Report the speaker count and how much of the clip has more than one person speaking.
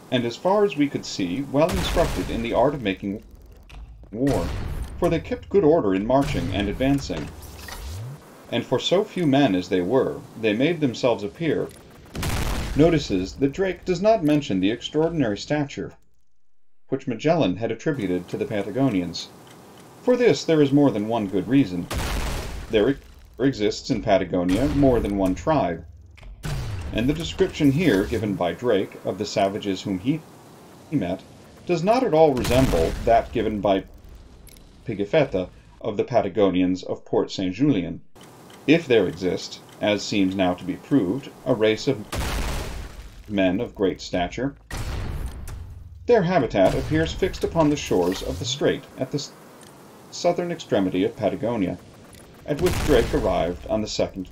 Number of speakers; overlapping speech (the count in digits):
1, no overlap